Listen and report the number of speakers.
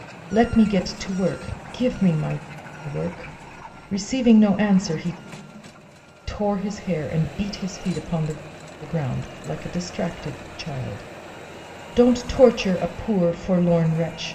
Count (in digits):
1